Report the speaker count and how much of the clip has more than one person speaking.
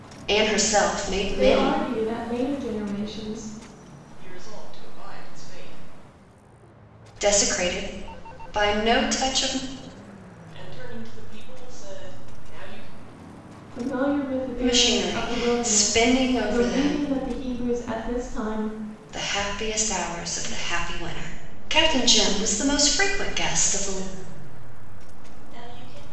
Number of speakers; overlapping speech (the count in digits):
3, about 22%